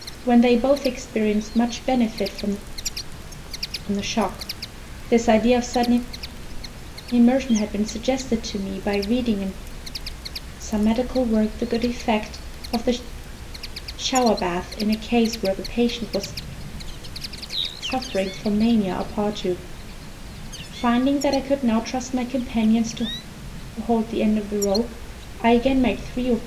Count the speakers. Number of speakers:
one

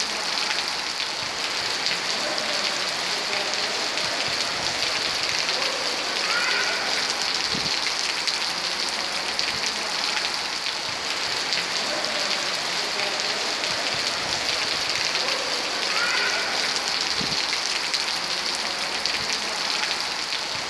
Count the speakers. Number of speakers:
zero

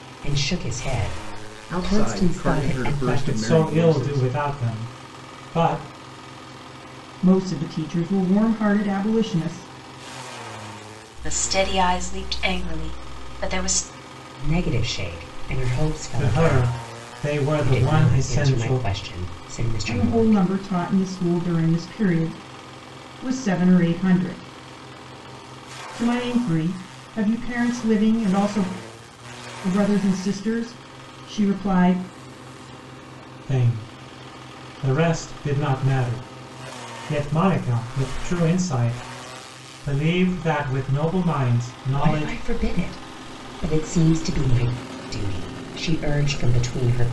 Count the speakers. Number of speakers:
five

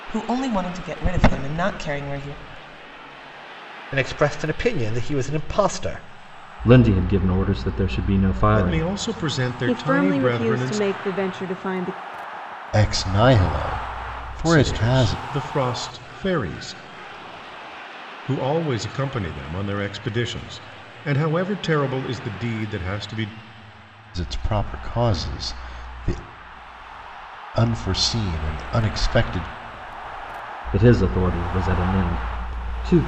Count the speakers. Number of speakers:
six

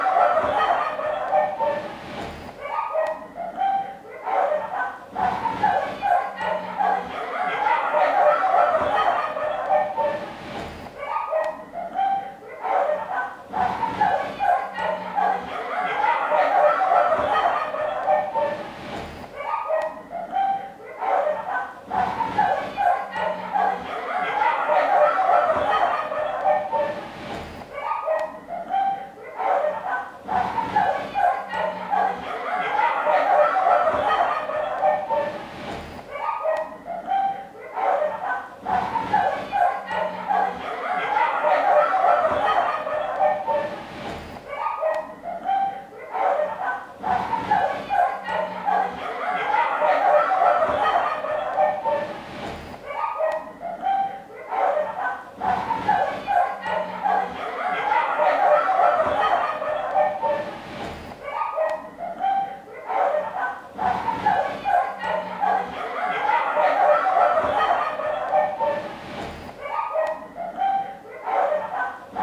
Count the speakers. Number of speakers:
zero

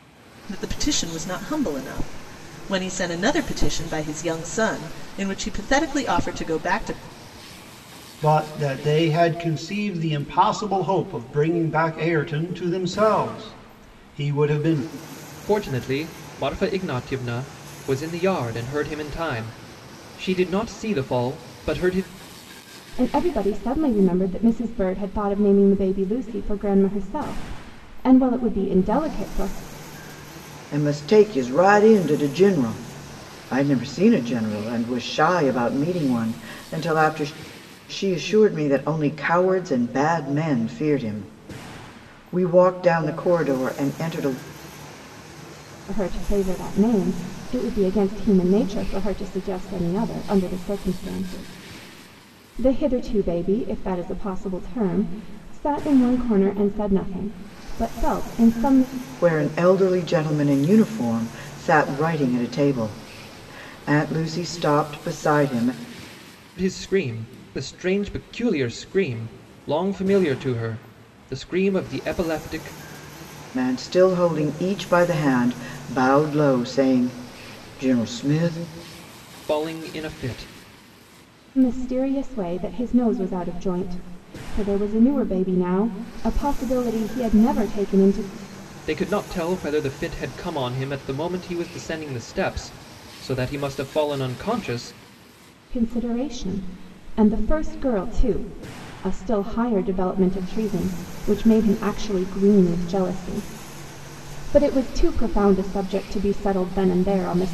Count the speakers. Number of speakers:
five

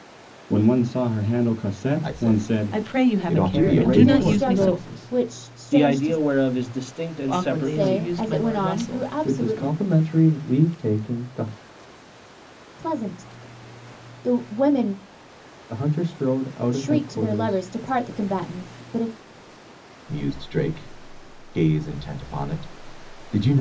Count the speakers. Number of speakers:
six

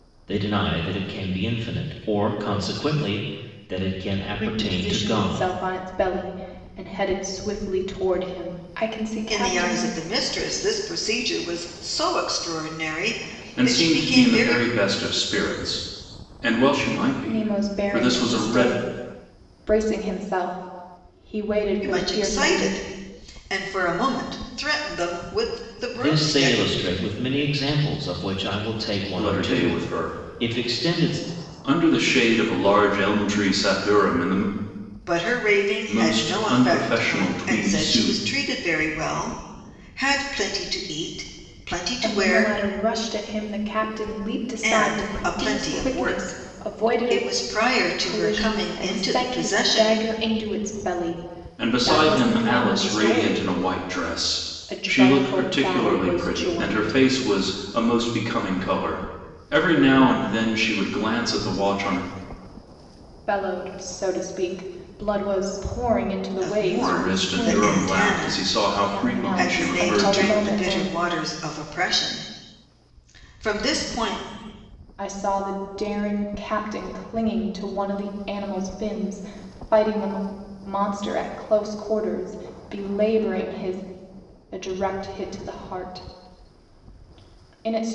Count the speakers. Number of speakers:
four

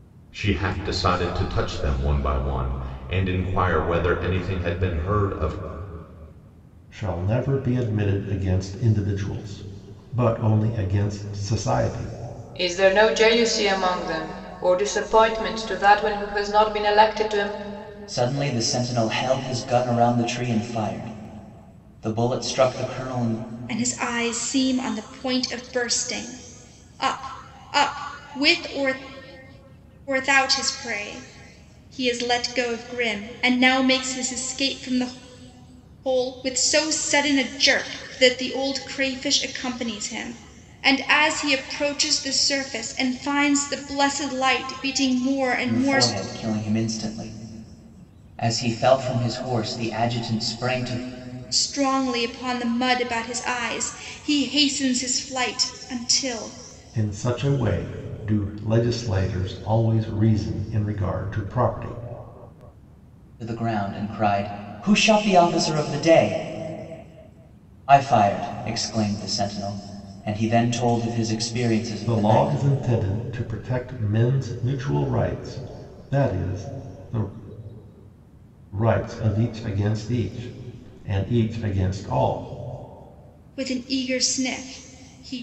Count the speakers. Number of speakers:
five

